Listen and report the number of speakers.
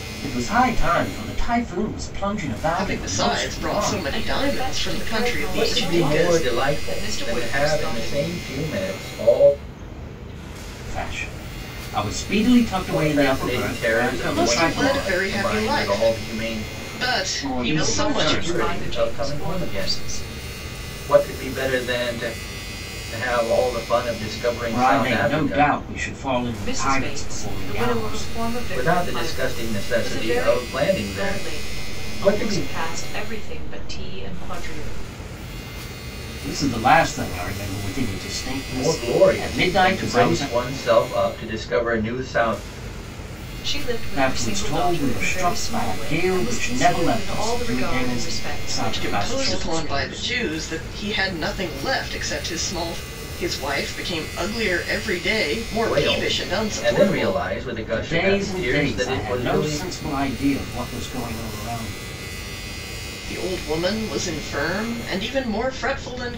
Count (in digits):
4